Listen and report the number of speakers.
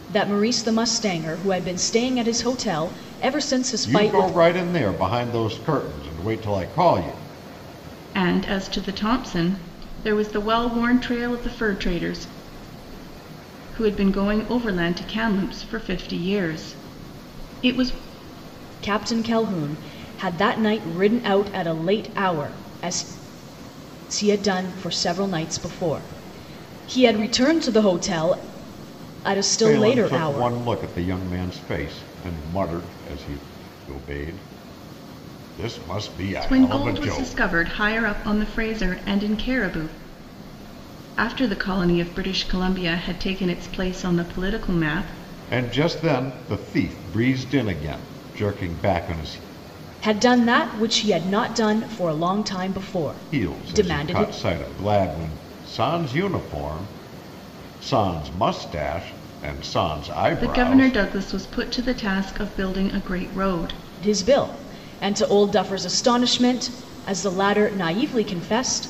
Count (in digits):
3